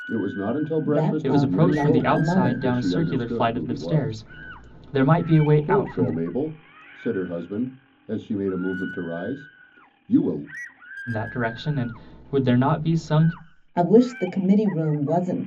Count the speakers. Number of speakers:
3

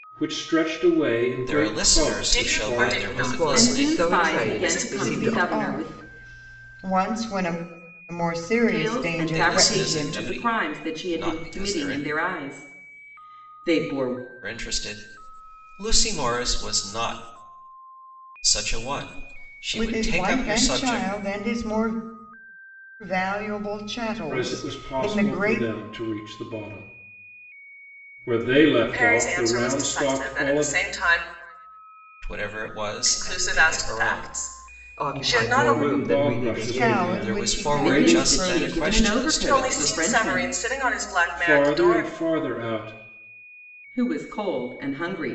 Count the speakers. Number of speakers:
6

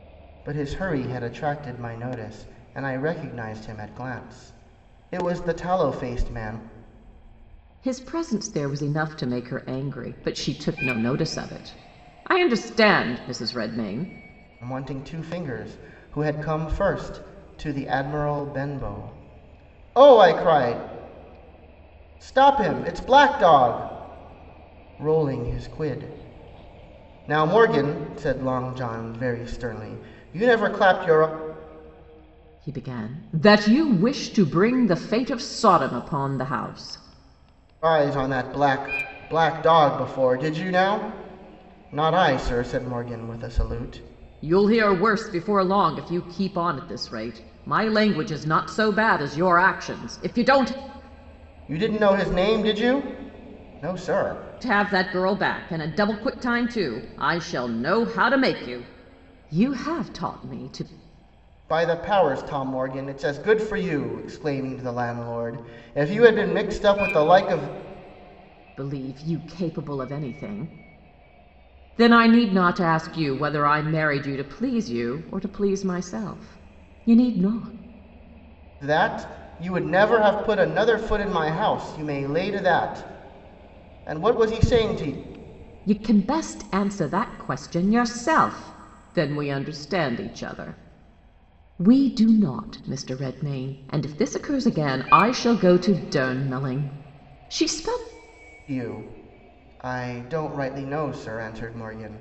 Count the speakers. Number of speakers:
2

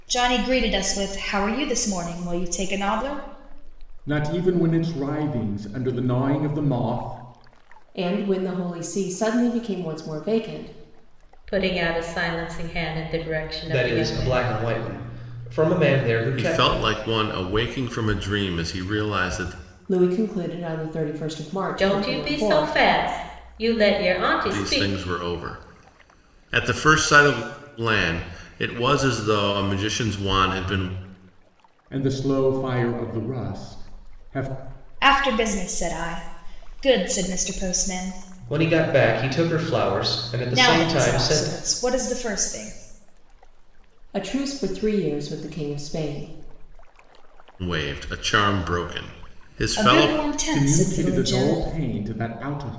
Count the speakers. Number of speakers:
6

